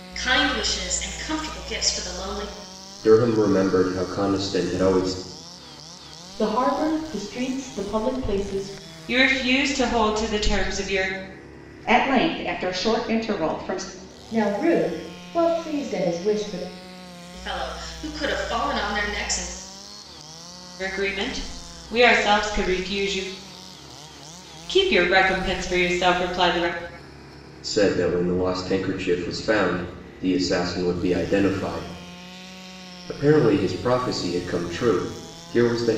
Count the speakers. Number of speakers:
six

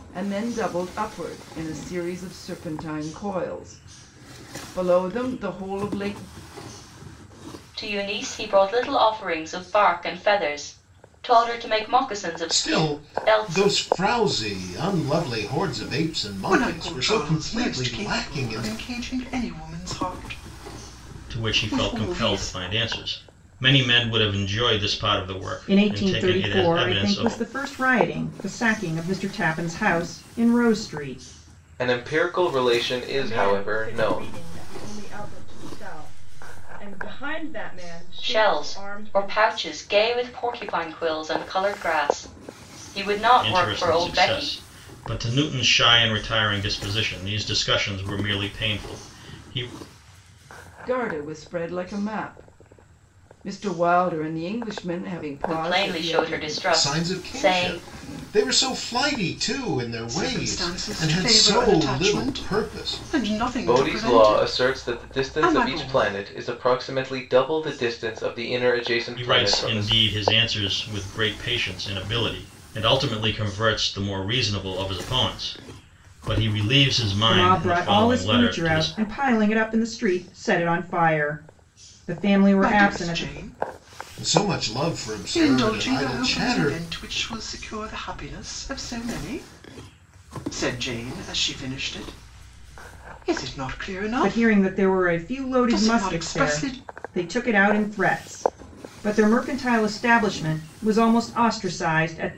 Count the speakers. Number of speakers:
eight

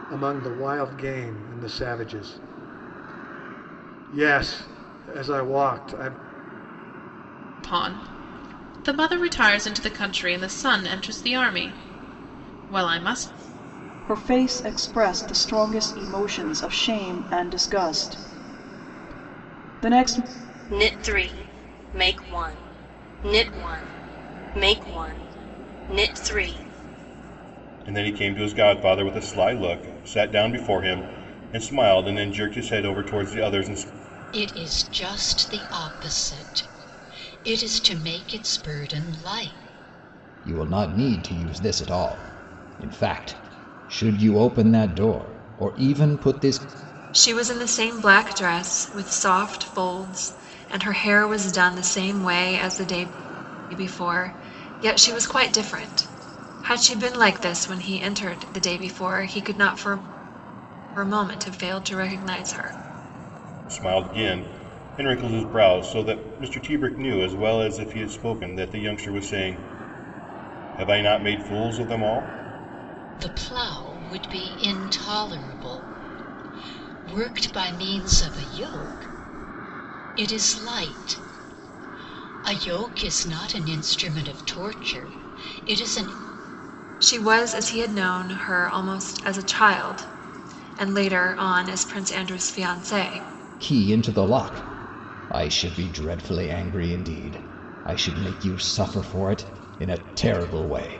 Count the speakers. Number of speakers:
eight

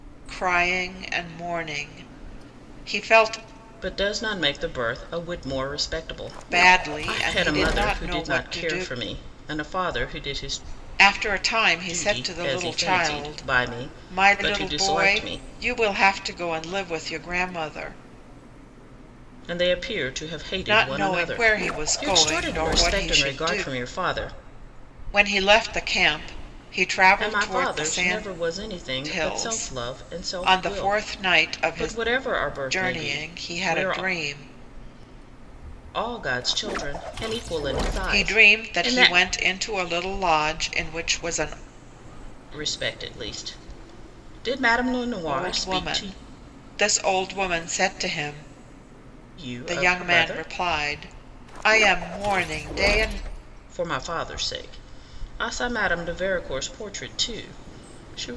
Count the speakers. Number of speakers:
two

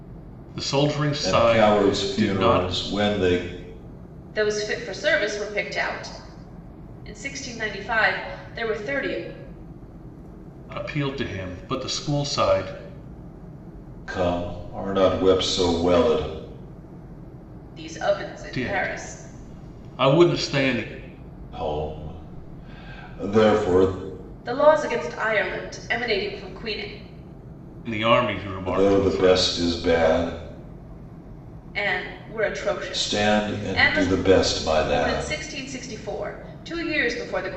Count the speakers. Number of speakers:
three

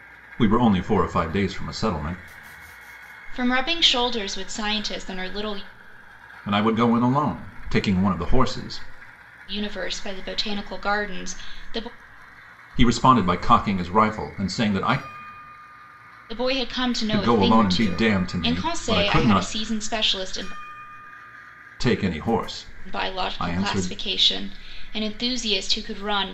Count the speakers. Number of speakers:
two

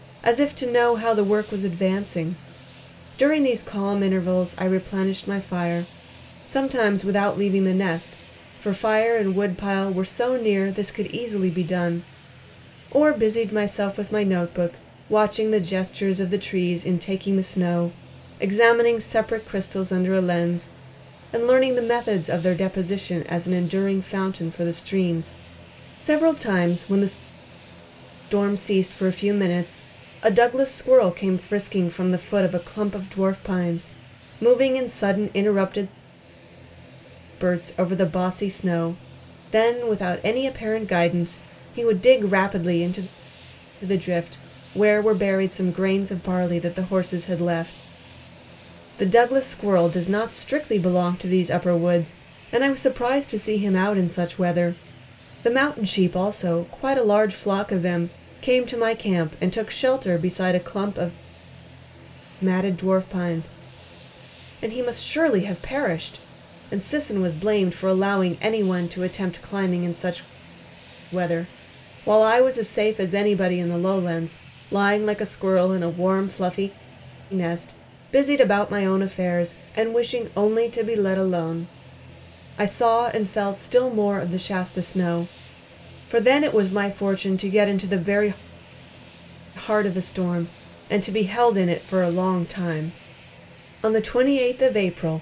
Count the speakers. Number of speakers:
one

